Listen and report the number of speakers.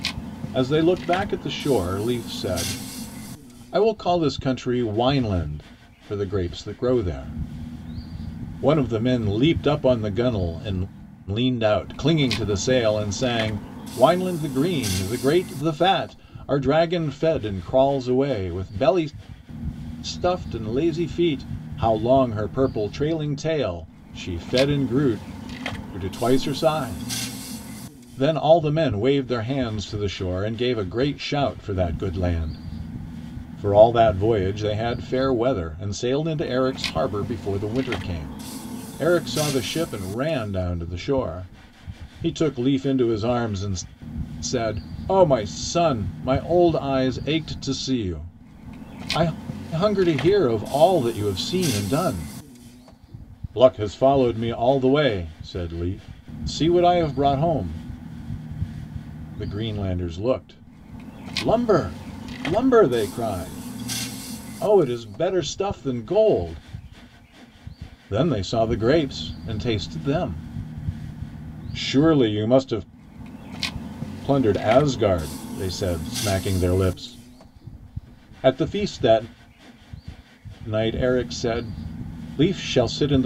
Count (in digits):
1